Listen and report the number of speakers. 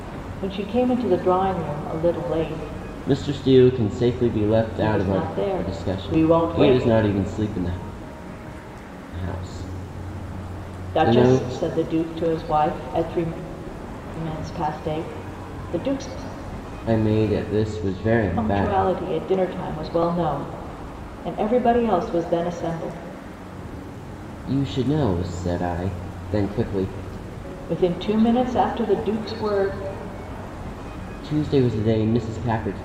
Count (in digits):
2